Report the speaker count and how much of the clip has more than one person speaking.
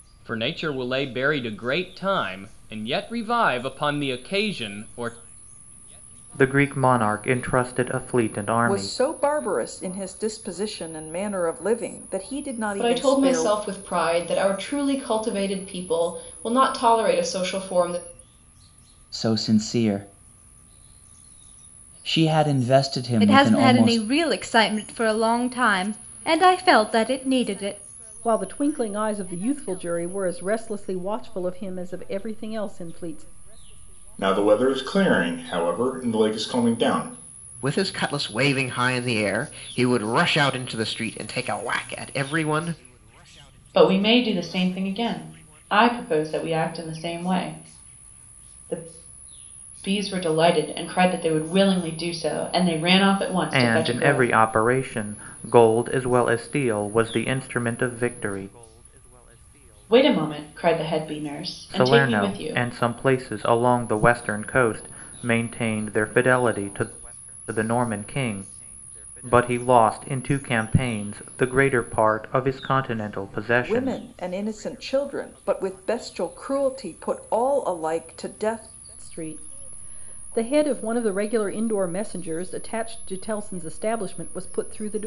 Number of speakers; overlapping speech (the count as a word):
ten, about 5%